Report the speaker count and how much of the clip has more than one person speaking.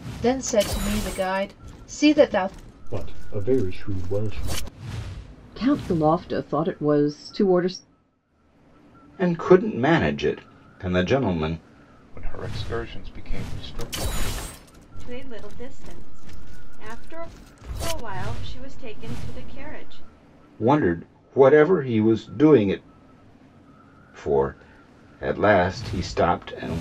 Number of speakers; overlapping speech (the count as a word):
six, no overlap